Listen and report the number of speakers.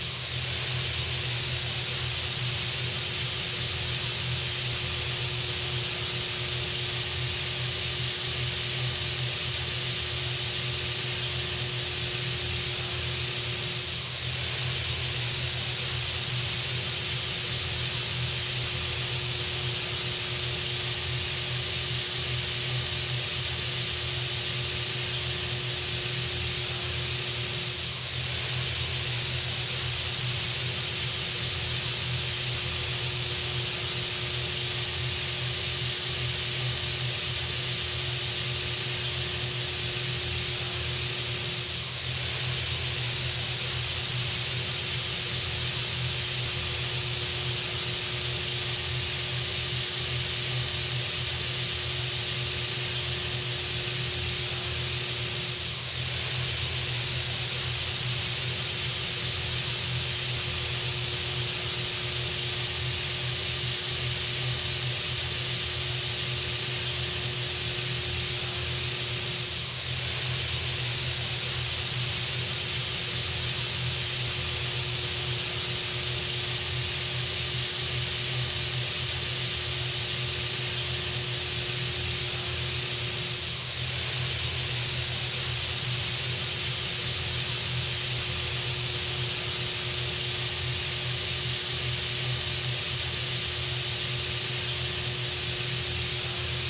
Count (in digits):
0